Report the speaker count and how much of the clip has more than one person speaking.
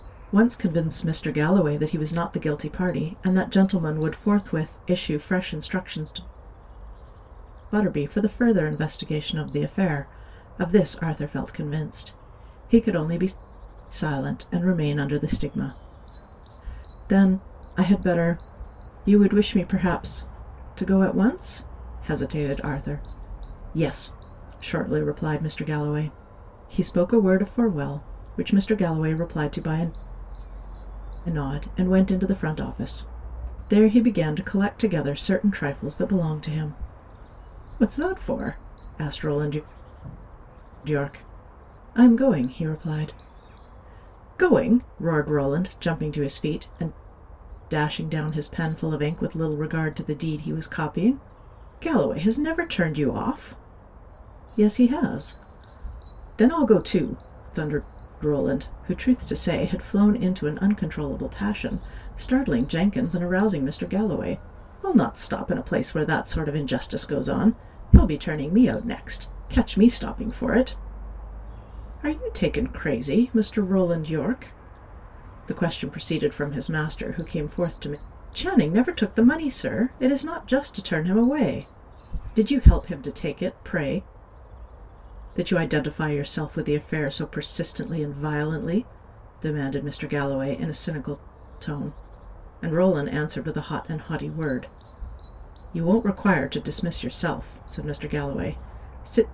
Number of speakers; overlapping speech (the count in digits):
1, no overlap